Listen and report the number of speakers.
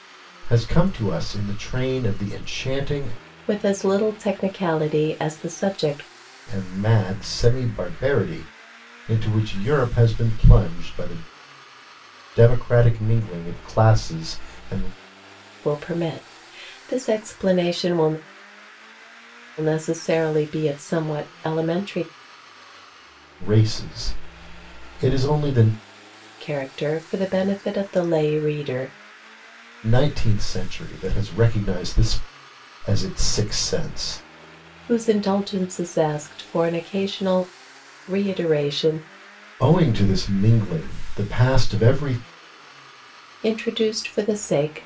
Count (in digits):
2